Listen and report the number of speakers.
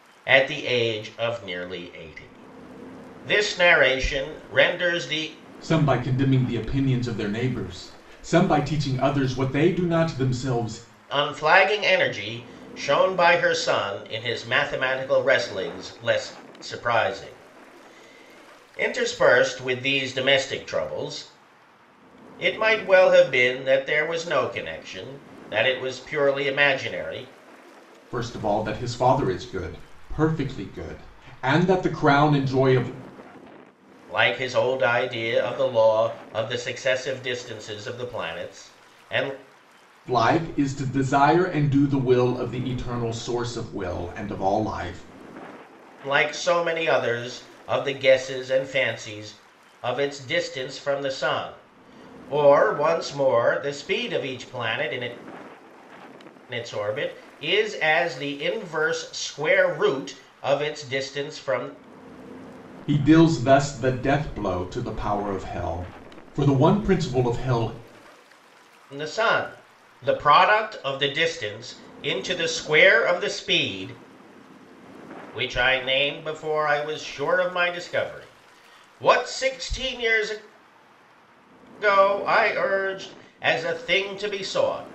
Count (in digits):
2